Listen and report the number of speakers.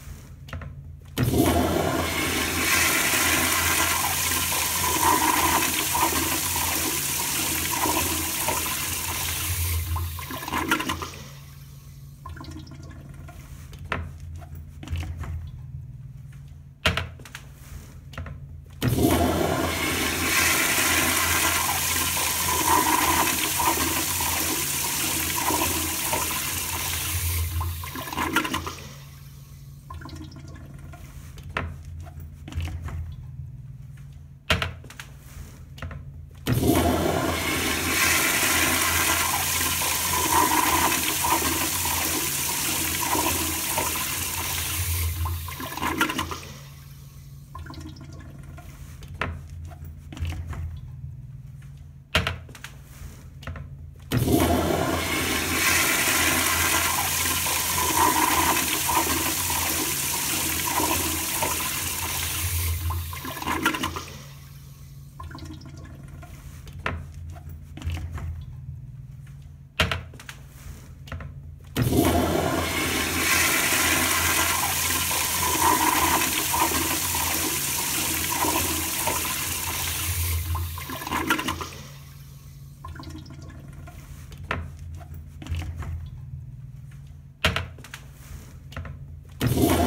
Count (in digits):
0